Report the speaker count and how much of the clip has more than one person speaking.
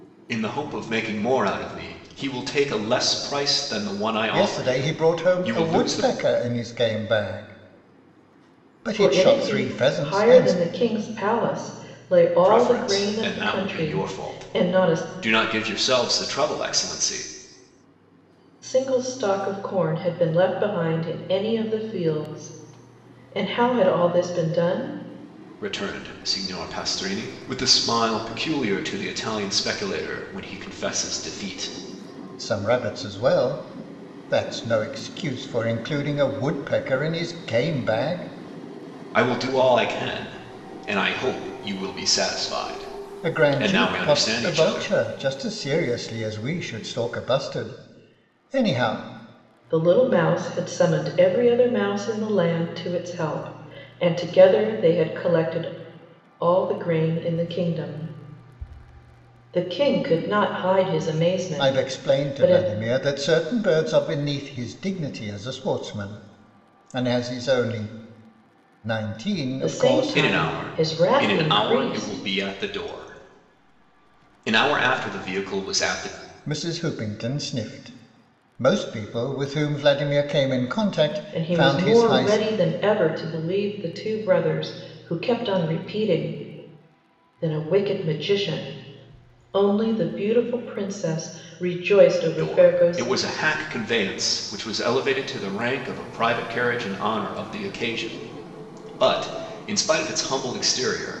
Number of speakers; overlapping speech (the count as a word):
three, about 14%